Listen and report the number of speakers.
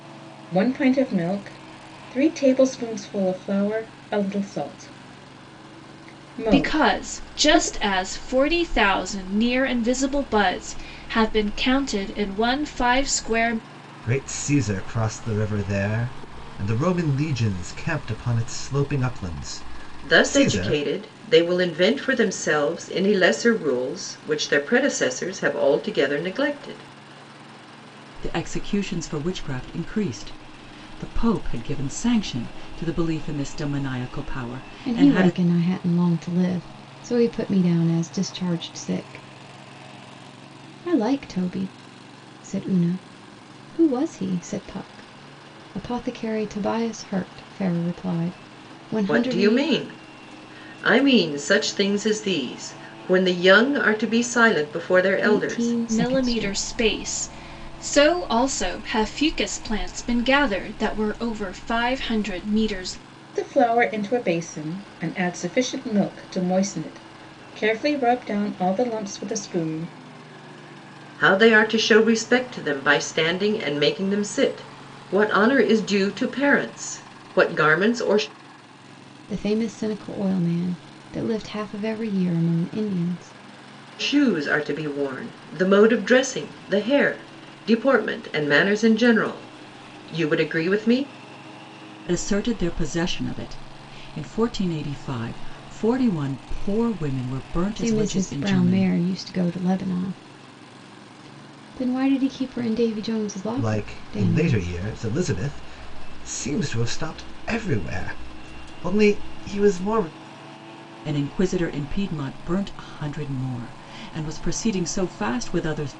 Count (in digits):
6